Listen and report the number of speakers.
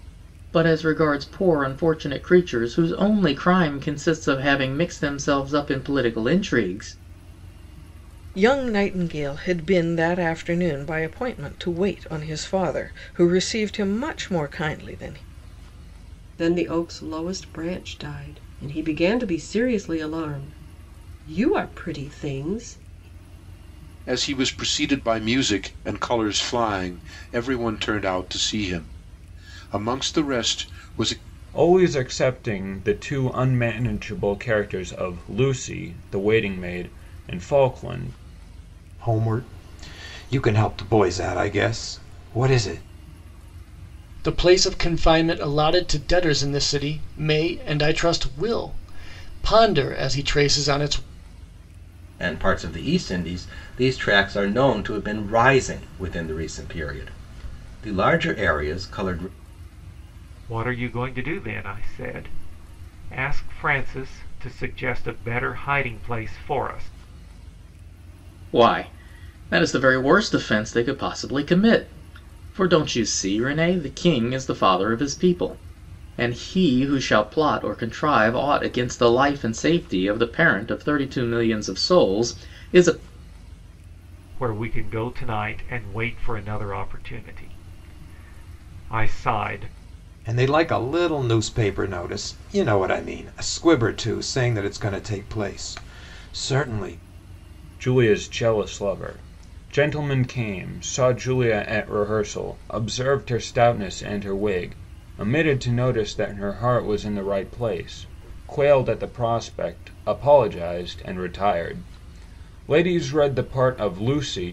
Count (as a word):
nine